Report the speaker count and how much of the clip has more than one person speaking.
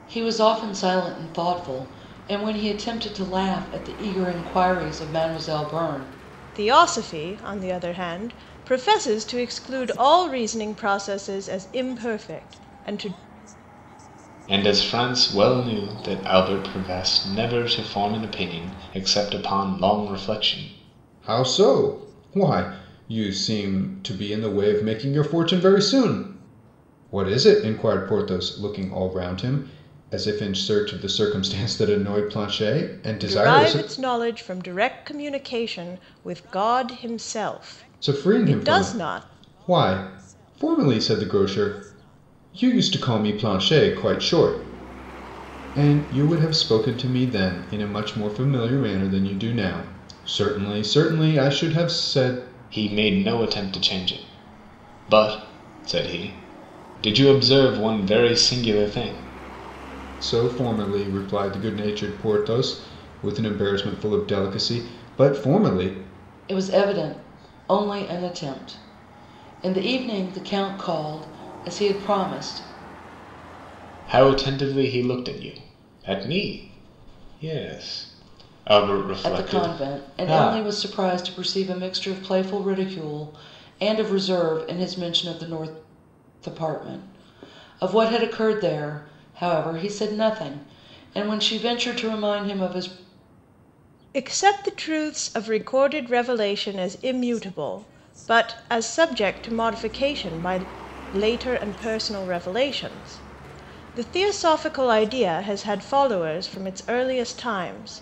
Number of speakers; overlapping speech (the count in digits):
4, about 3%